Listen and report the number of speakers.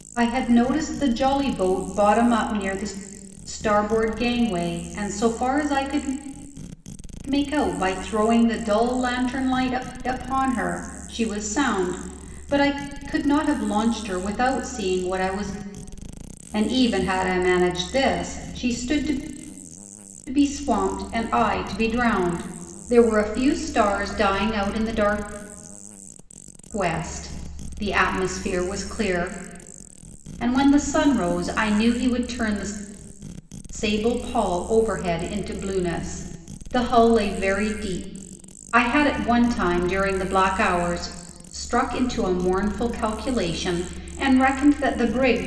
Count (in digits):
1